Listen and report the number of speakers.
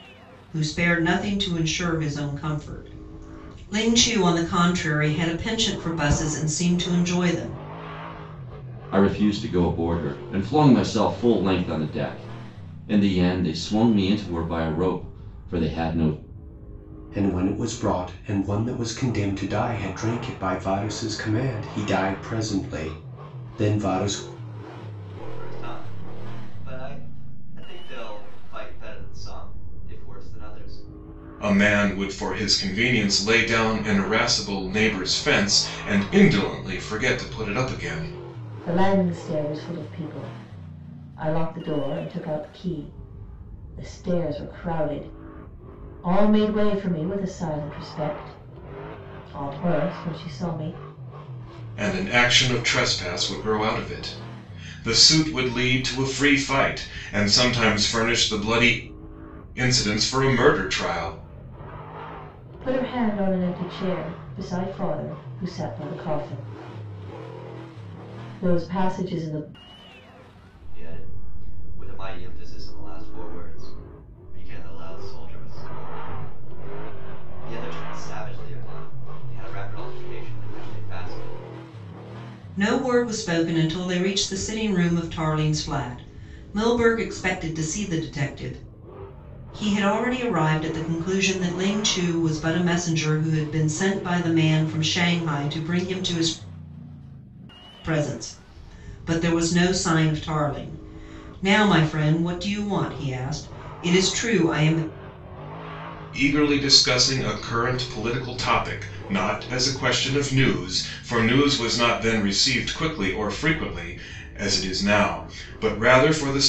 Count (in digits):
6